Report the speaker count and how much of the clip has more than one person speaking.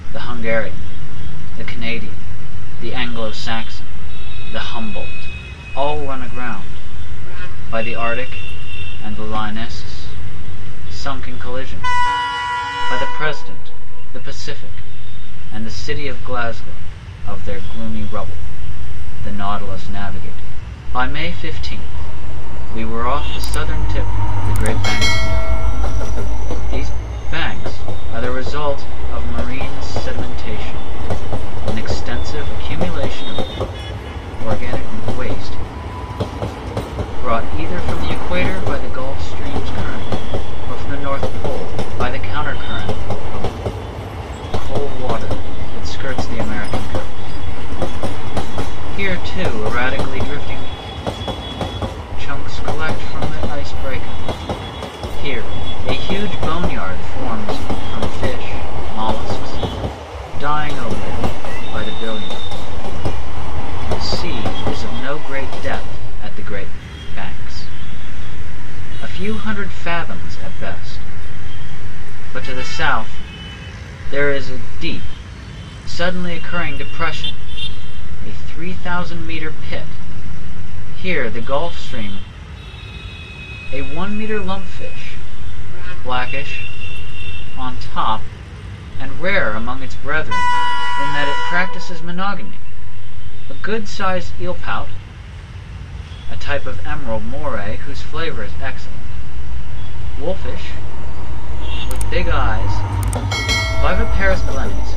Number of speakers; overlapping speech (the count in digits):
1, no overlap